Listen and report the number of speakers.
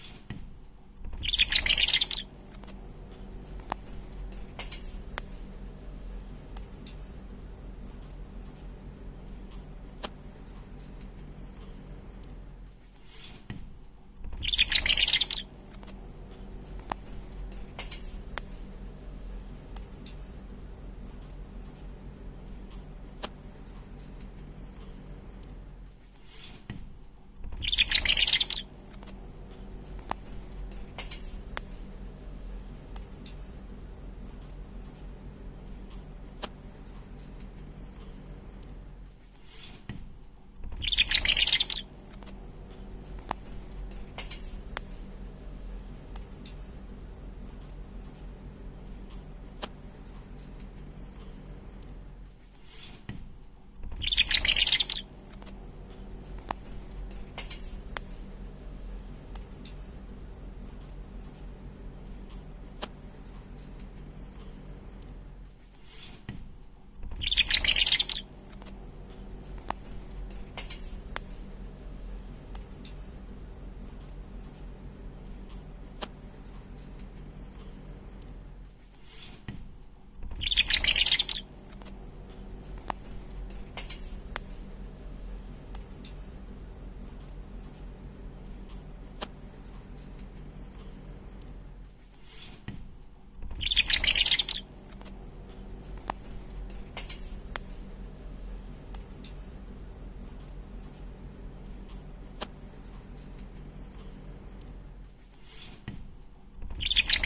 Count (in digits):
0